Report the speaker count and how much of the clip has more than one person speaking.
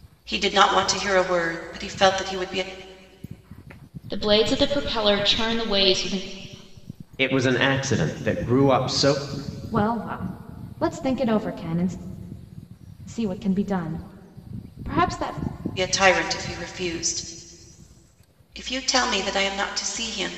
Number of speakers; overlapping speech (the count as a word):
four, no overlap